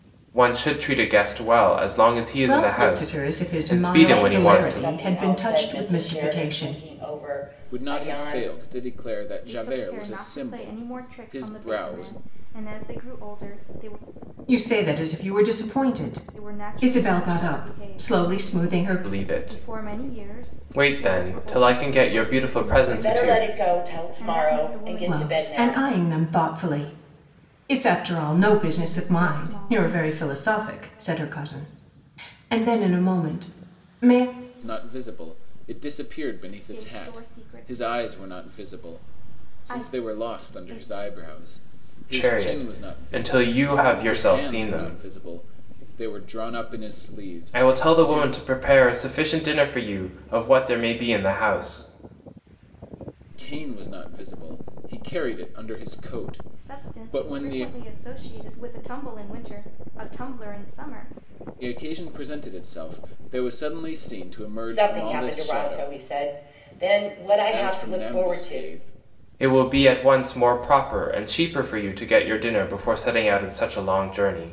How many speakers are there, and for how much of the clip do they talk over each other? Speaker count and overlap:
5, about 39%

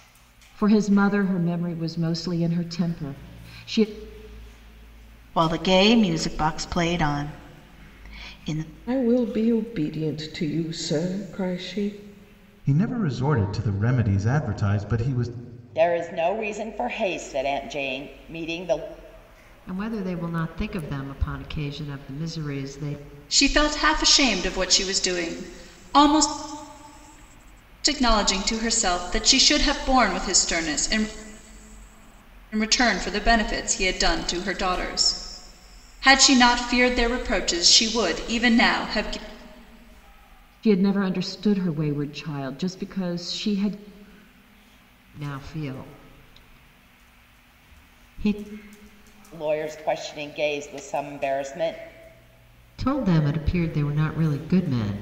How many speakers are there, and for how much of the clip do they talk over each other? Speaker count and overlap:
7, no overlap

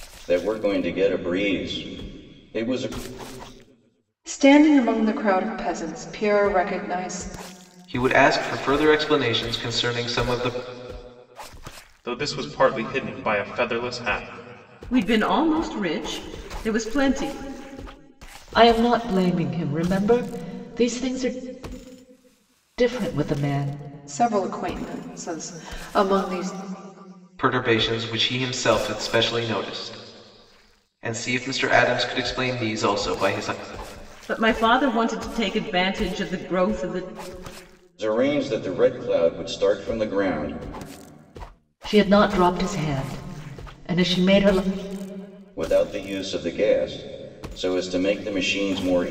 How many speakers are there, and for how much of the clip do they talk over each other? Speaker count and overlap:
6, no overlap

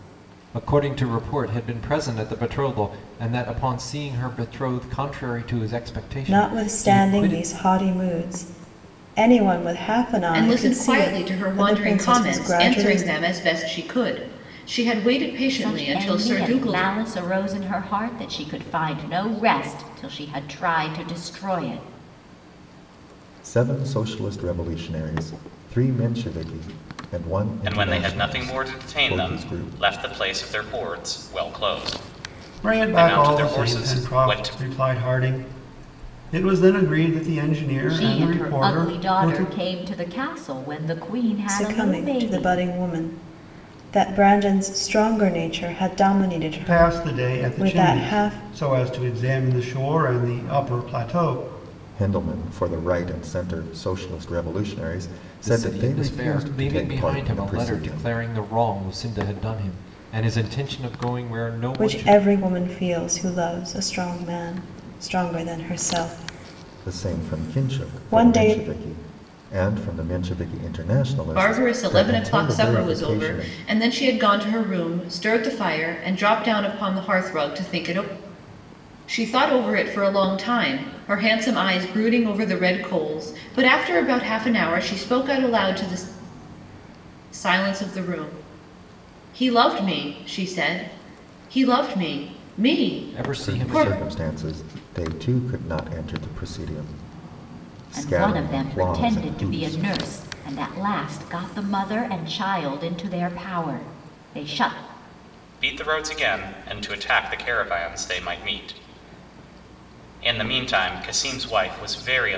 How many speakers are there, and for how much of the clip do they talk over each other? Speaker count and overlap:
7, about 22%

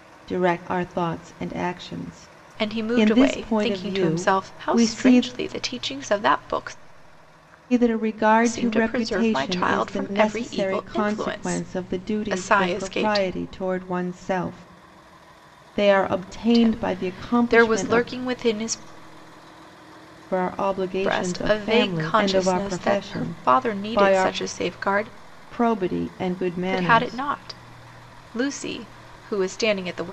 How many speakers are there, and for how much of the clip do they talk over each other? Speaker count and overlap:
2, about 43%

